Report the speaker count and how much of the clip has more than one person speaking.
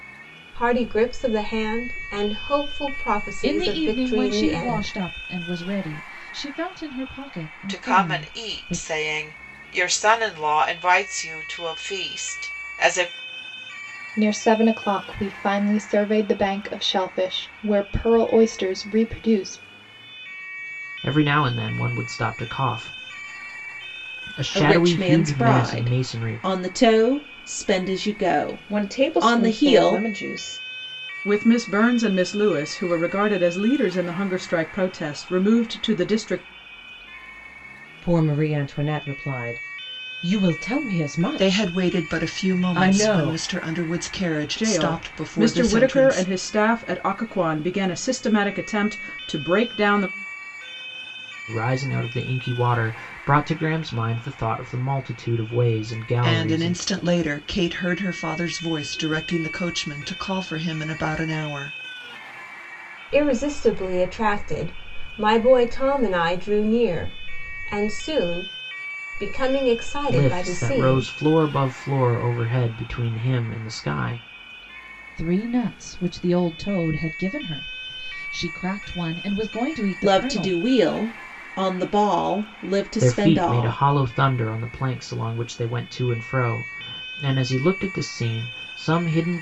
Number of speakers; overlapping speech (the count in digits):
10, about 15%